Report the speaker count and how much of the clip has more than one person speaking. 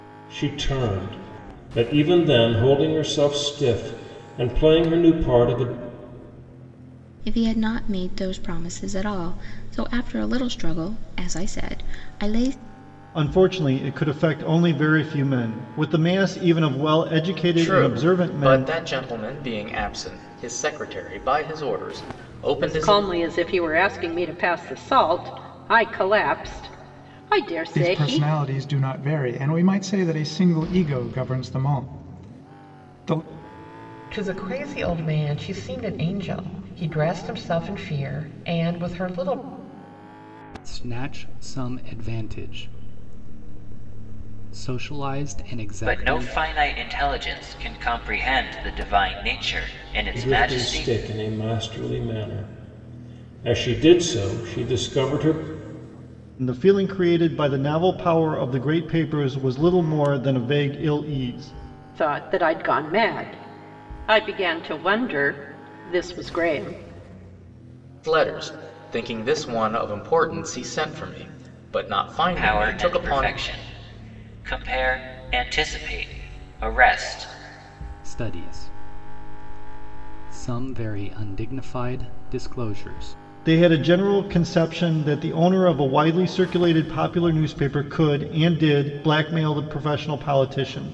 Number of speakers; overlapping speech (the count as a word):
nine, about 5%